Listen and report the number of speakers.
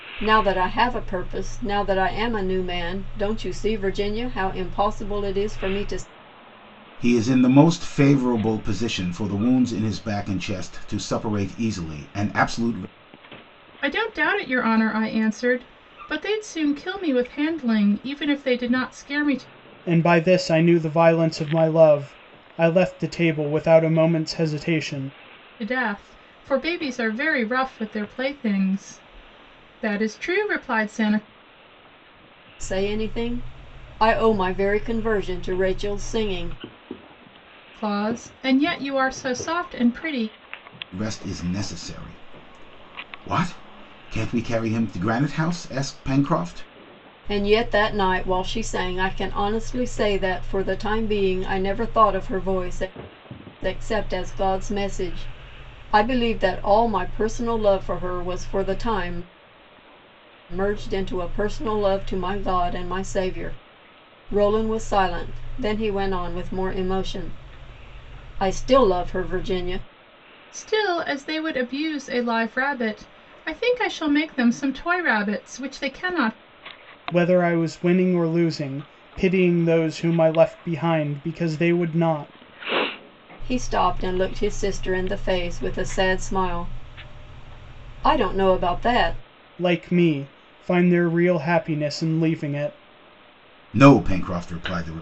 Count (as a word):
four